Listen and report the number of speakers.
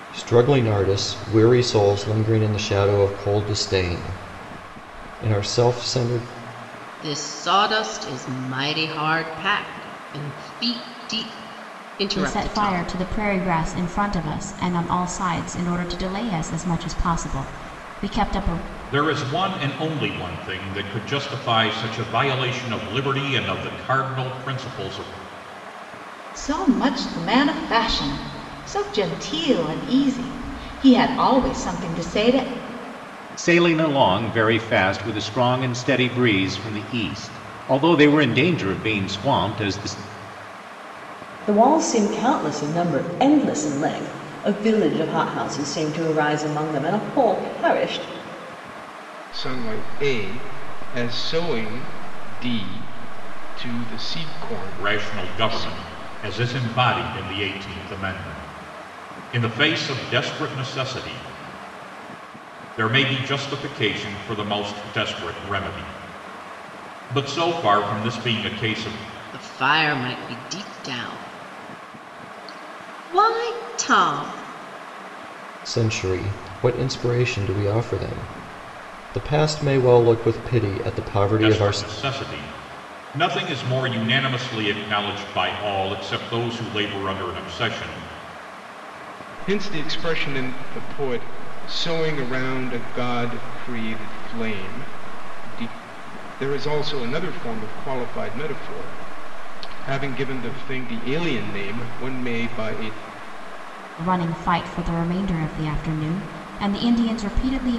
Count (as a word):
eight